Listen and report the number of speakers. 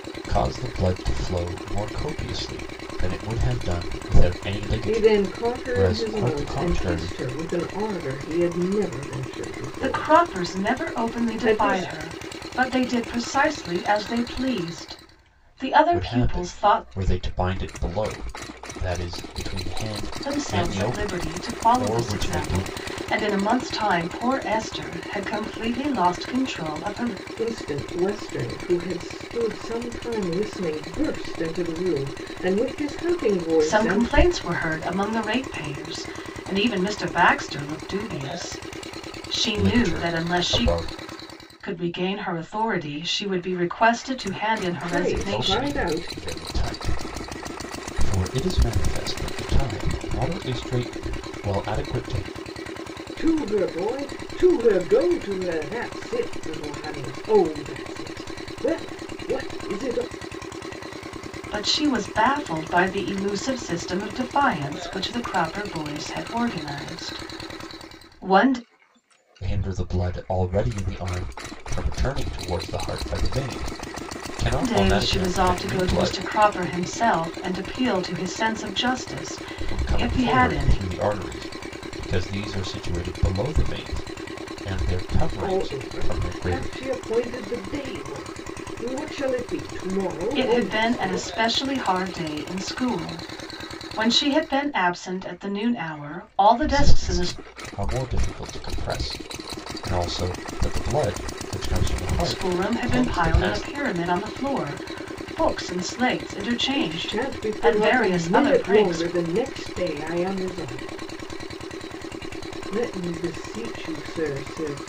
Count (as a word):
three